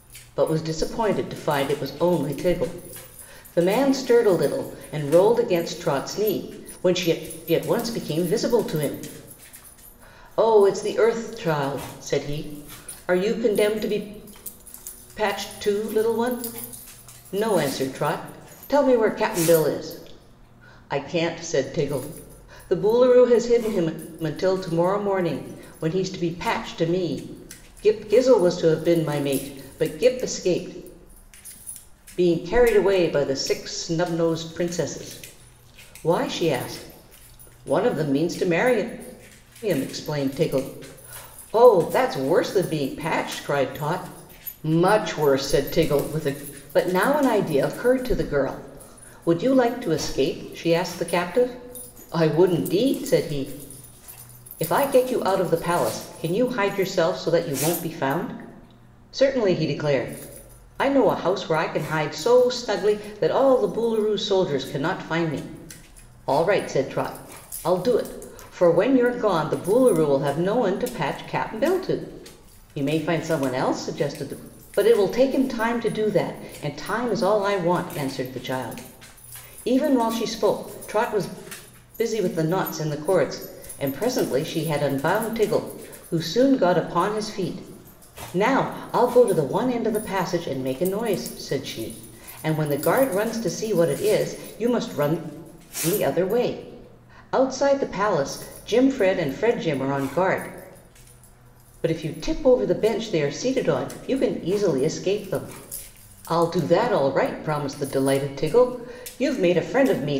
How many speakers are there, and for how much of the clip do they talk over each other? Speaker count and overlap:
one, no overlap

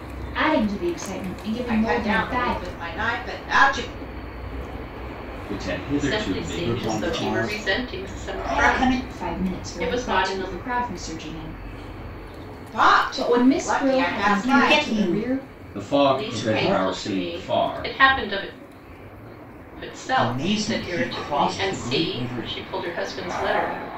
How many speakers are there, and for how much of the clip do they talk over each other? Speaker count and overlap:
five, about 52%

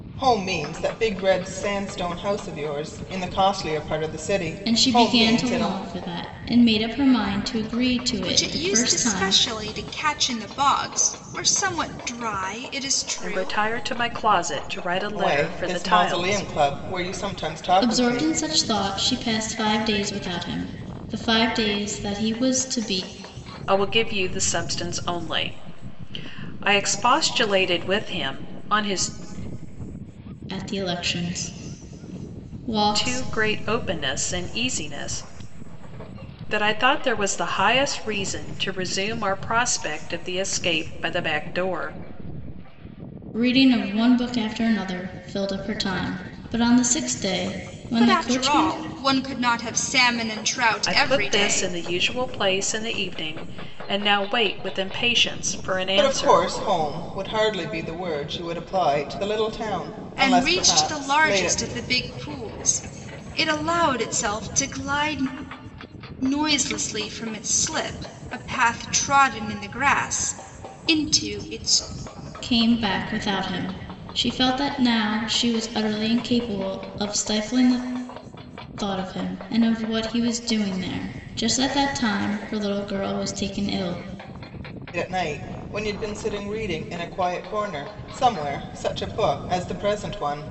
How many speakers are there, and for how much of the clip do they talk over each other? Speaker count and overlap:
four, about 10%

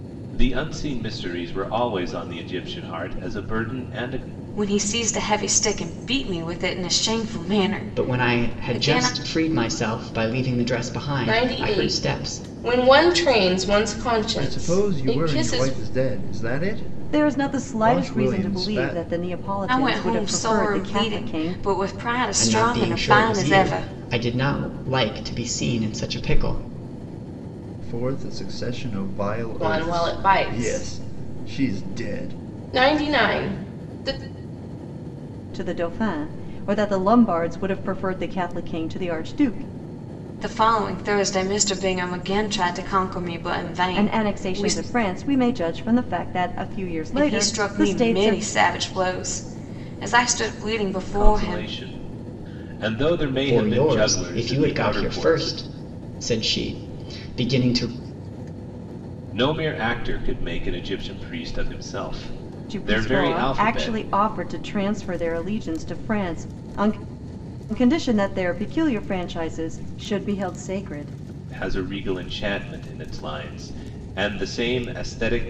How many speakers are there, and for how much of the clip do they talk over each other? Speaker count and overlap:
six, about 25%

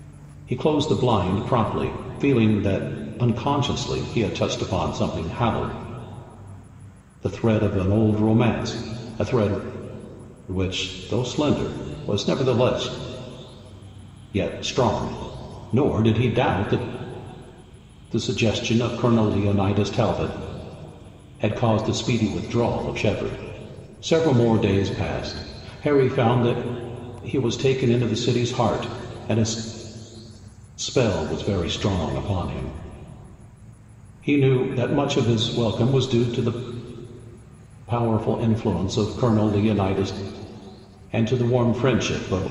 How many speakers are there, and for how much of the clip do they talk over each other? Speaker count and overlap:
one, no overlap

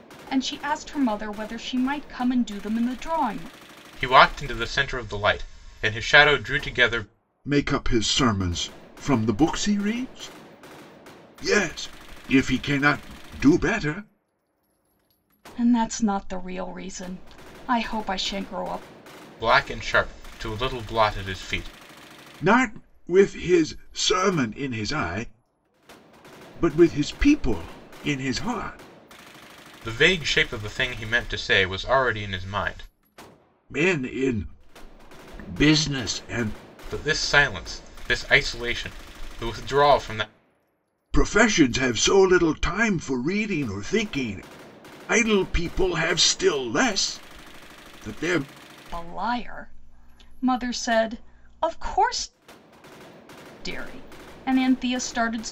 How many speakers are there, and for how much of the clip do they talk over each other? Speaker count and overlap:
three, no overlap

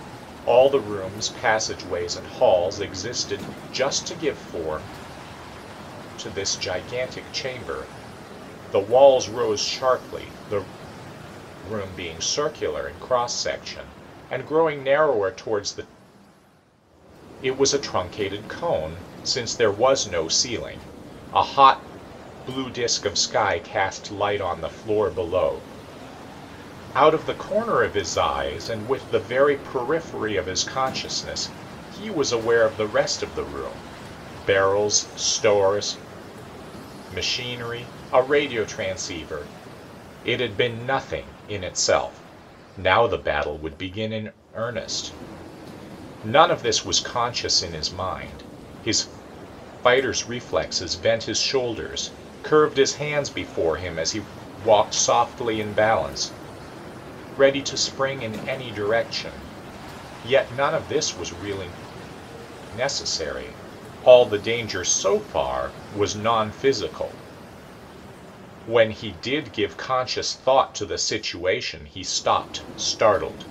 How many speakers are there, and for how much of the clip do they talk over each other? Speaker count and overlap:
one, no overlap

